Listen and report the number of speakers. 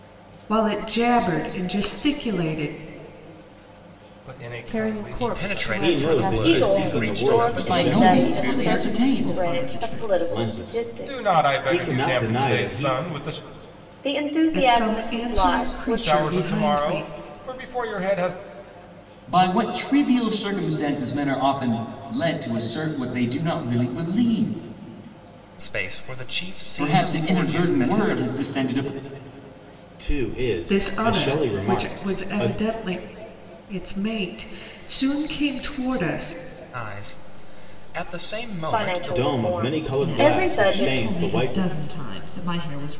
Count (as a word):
eight